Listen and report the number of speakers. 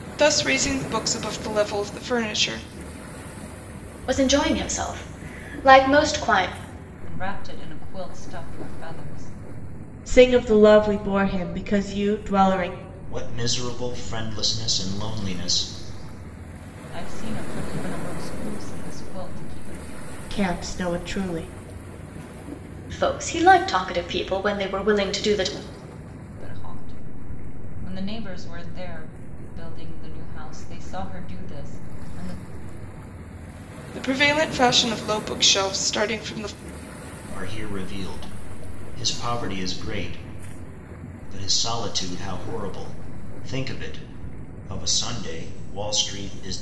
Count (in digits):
5